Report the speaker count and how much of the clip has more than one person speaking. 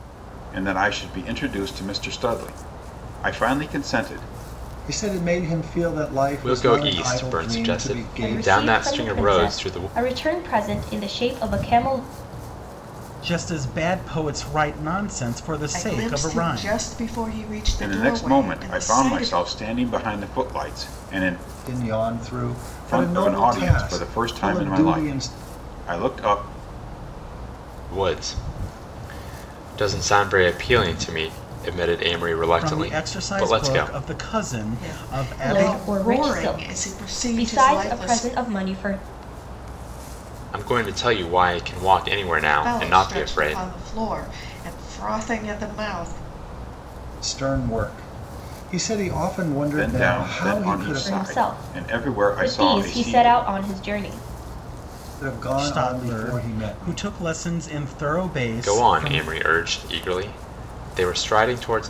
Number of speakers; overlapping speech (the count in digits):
6, about 34%